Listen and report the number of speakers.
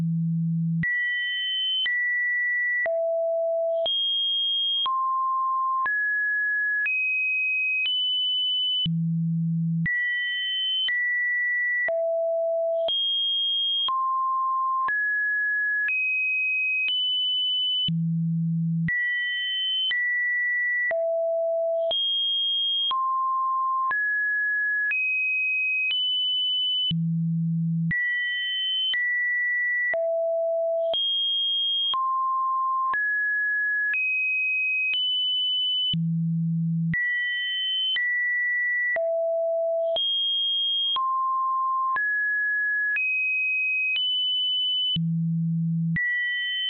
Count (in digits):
0